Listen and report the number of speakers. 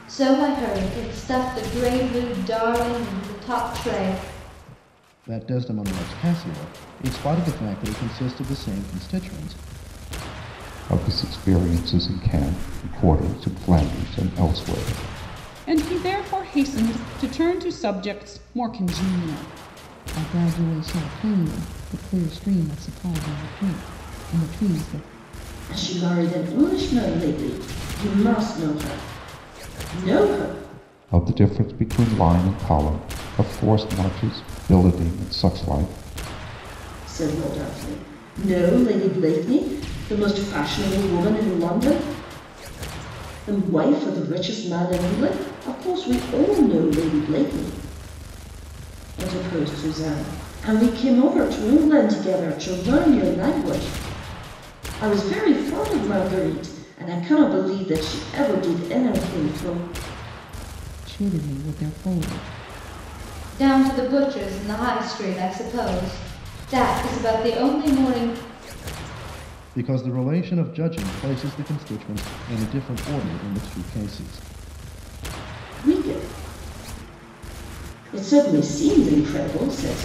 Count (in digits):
6